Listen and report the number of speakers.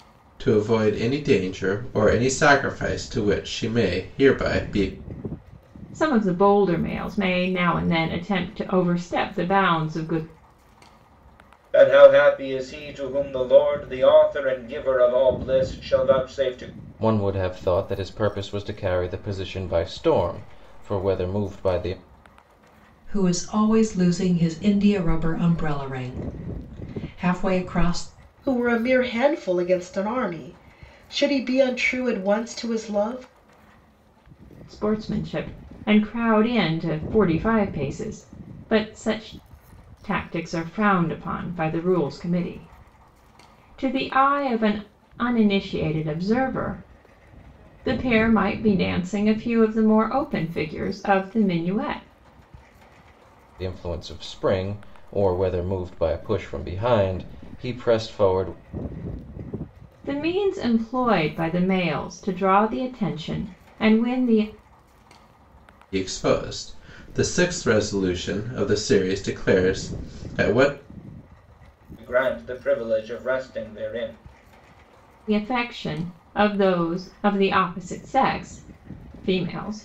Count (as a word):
six